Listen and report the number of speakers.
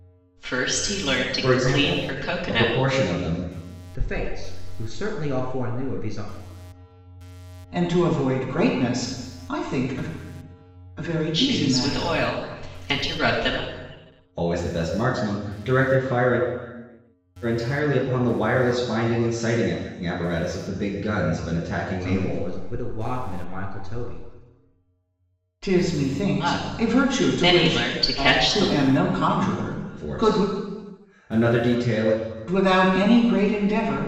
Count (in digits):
4